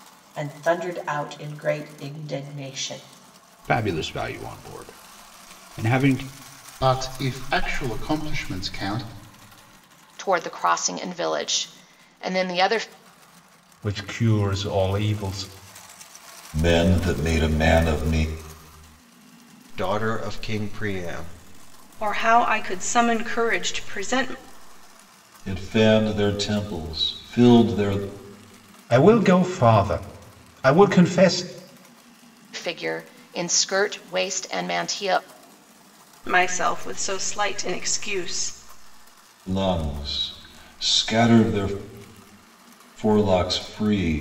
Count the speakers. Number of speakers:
8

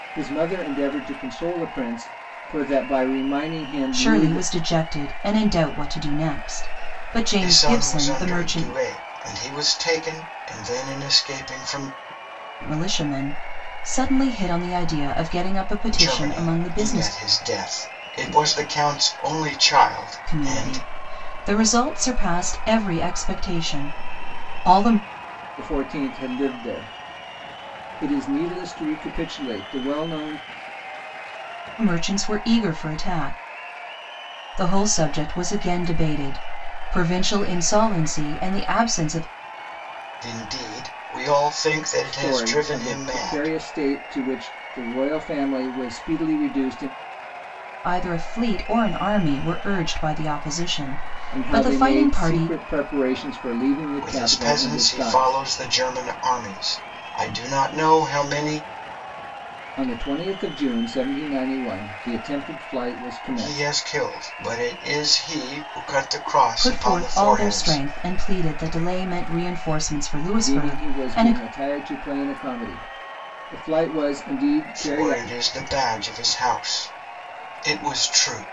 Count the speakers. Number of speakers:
3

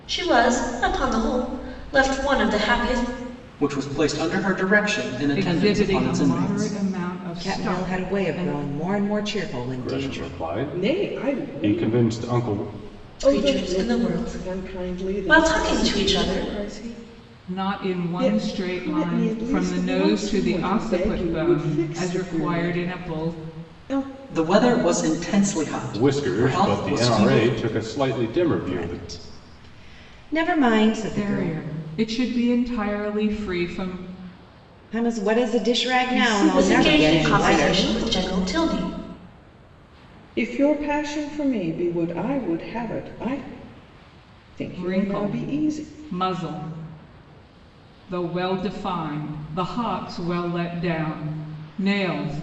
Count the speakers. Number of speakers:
6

